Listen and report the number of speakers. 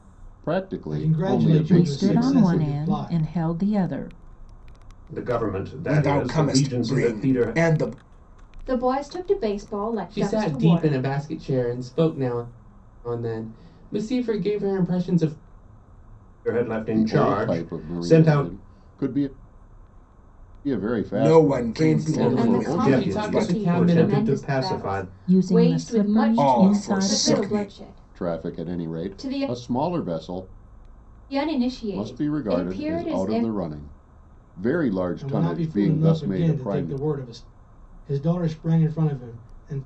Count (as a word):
seven